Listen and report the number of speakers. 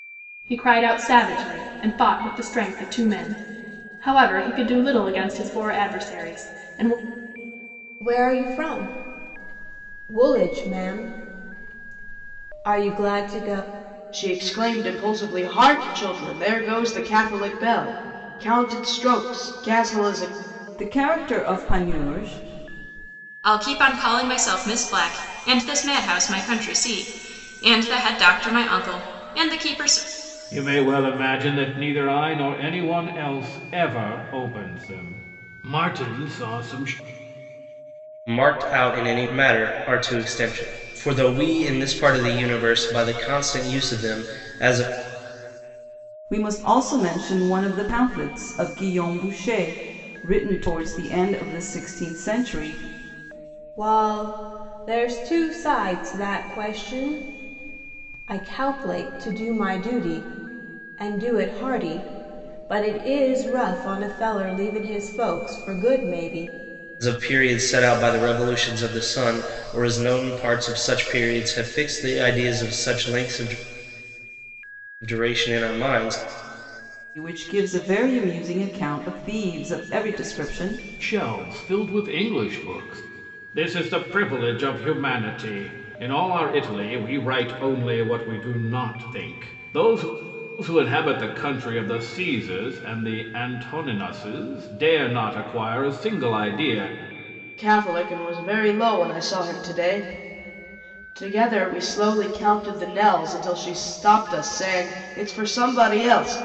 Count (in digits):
7